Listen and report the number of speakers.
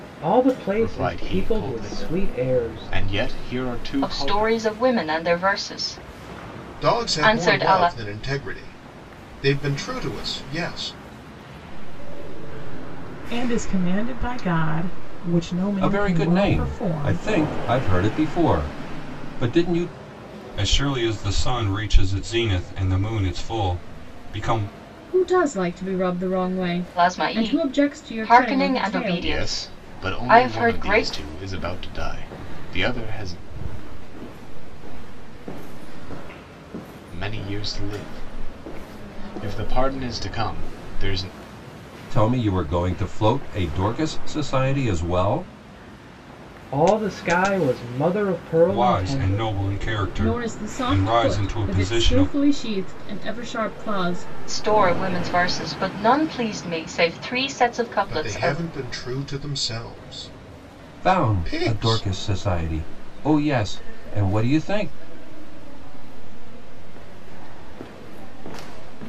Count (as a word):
nine